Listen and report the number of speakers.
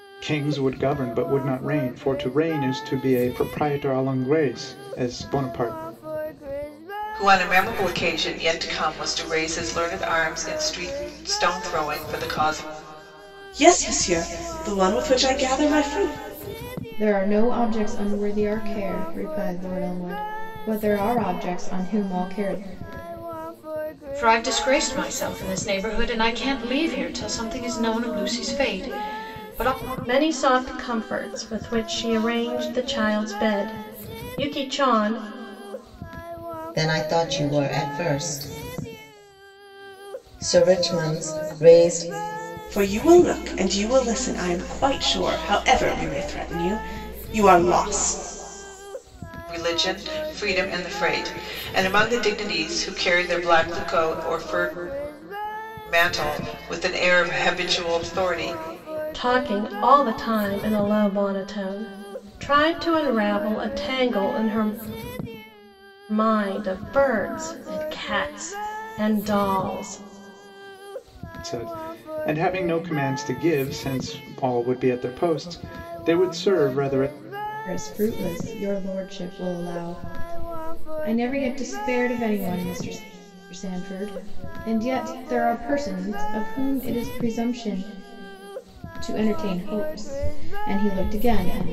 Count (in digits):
7